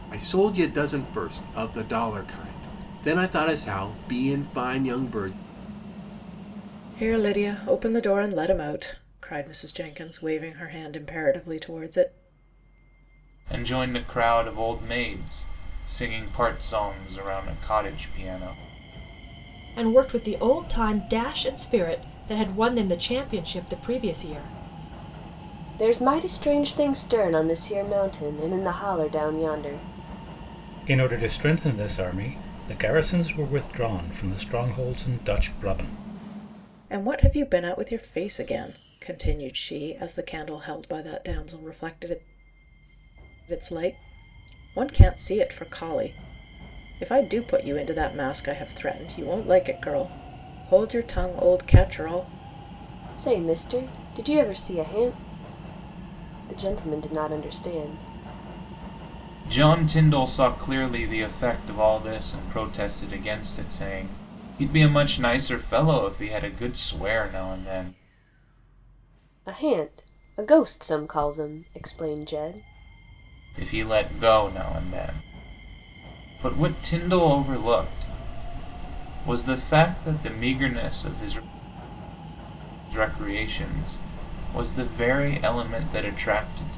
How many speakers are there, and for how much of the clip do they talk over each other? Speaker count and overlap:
6, no overlap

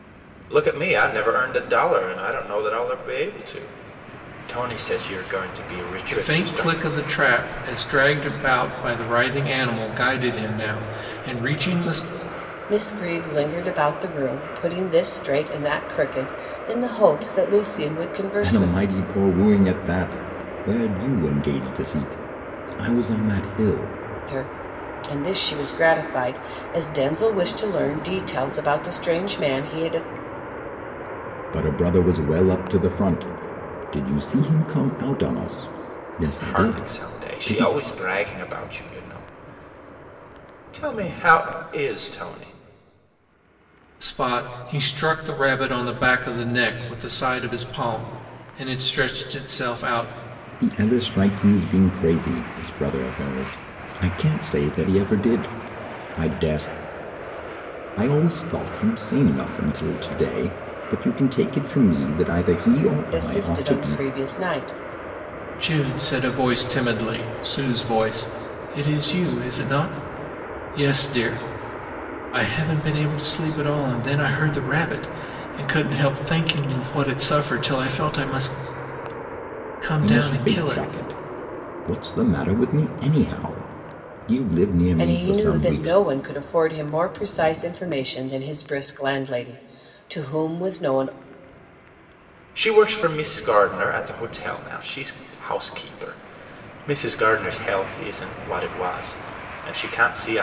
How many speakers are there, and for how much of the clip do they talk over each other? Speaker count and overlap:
4, about 5%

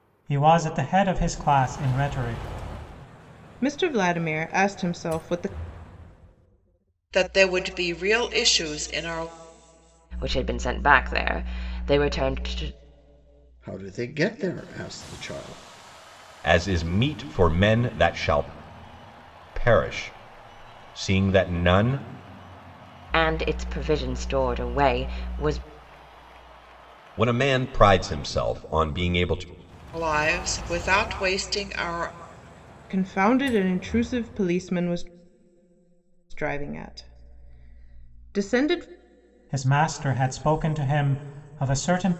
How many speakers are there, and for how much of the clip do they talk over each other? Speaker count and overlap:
6, no overlap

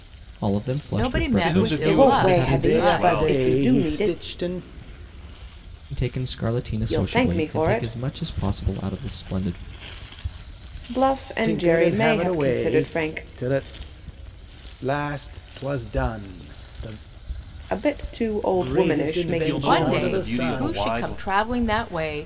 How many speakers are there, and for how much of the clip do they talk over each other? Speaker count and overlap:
5, about 40%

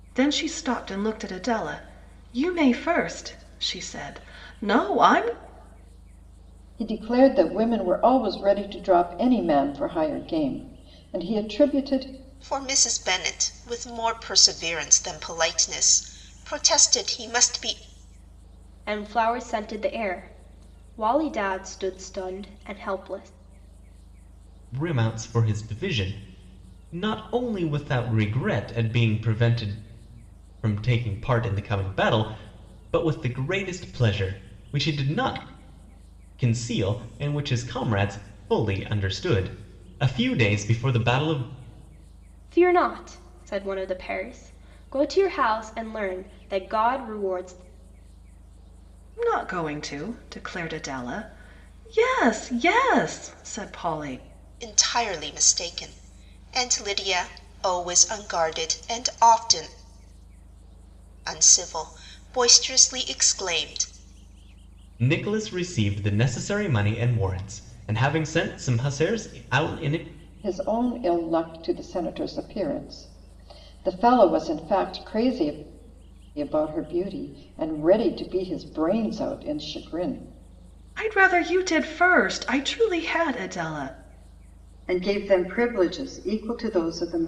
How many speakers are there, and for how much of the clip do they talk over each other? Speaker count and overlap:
5, no overlap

